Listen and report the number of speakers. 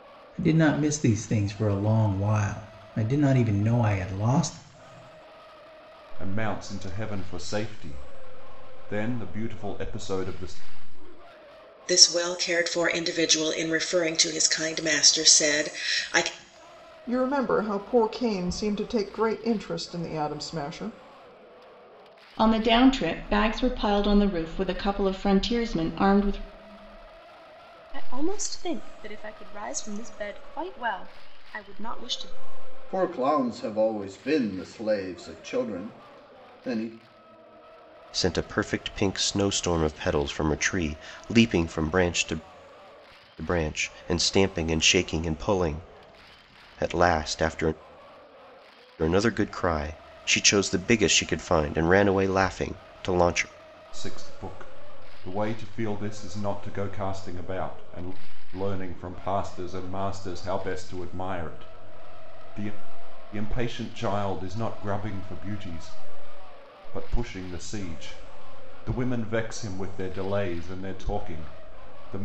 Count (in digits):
8